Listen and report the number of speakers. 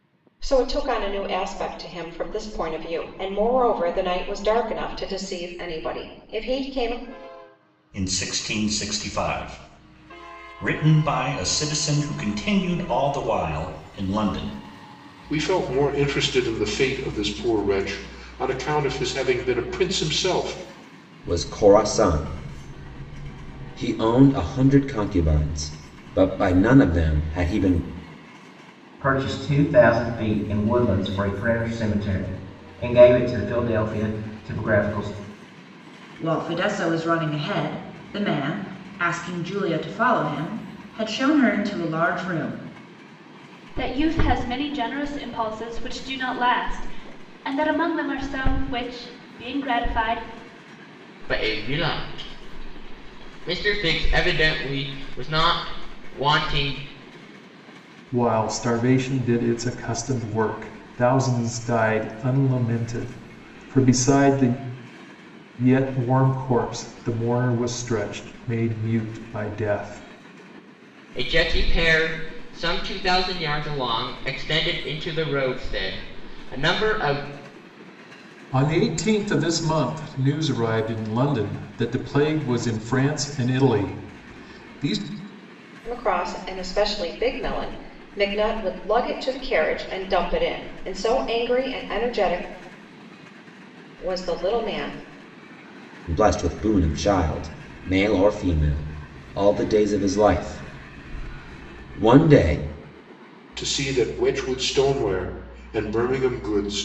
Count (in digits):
9